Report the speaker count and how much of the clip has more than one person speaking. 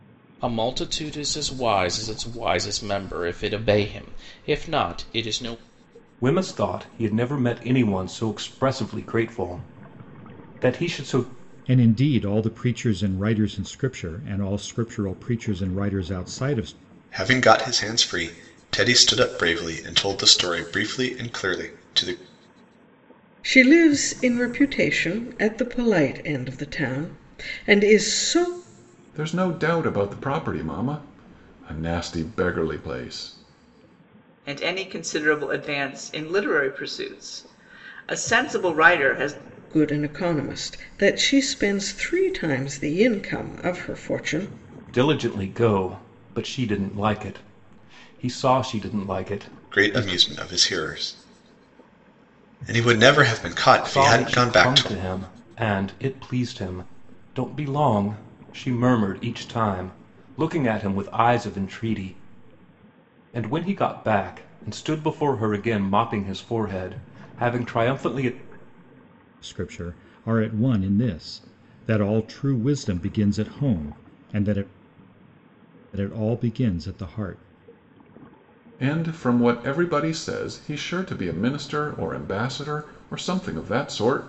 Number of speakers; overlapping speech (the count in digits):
7, about 2%